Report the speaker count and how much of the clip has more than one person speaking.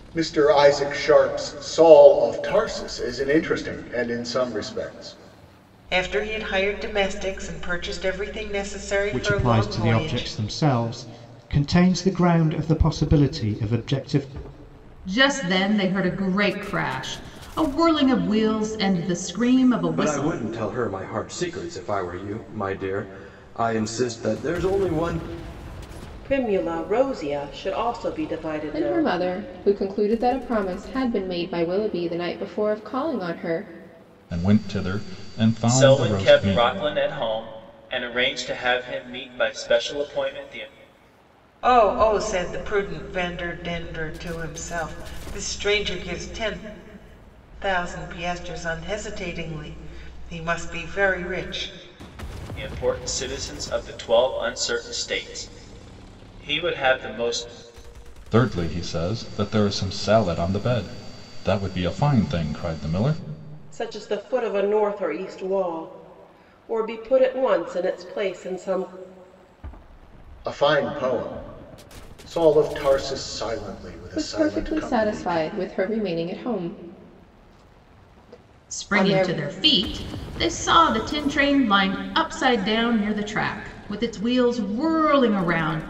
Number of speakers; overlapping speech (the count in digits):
9, about 6%